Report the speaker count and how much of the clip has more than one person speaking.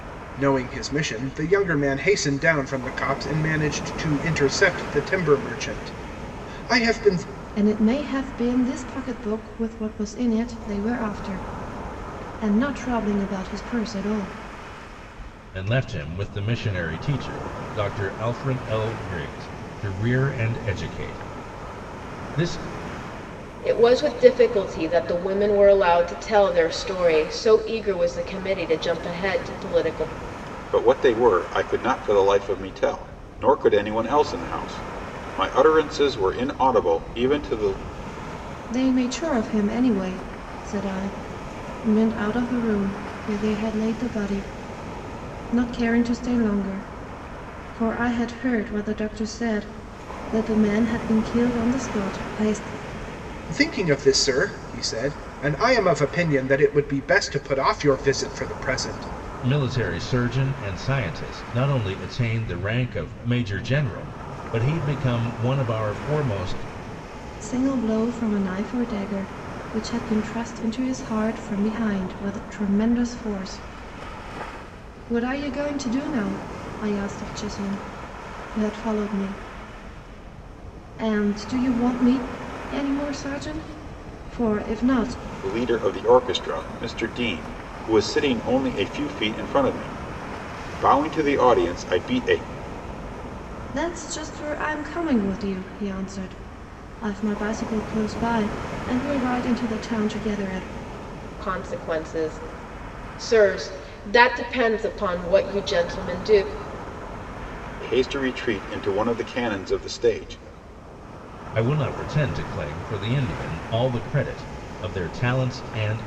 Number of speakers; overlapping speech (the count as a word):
five, no overlap